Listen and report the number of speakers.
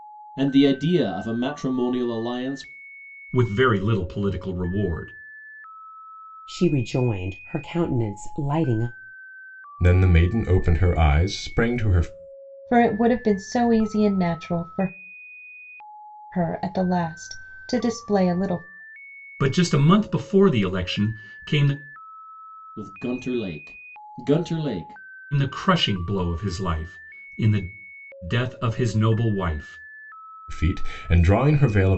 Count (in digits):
5